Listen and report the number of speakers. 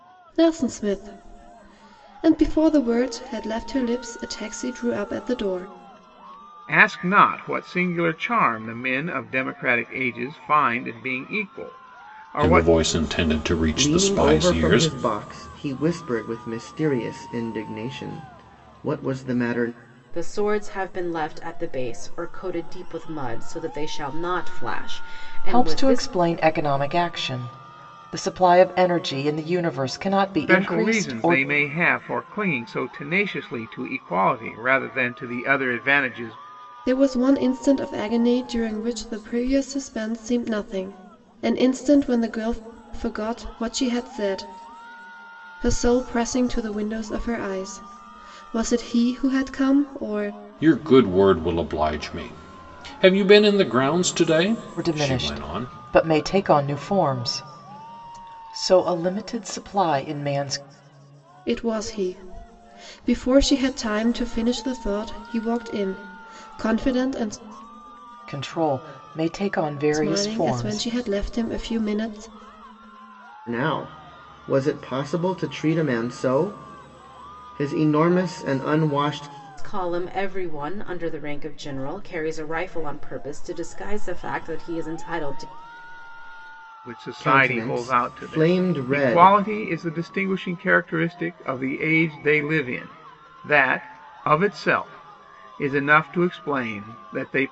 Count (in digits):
6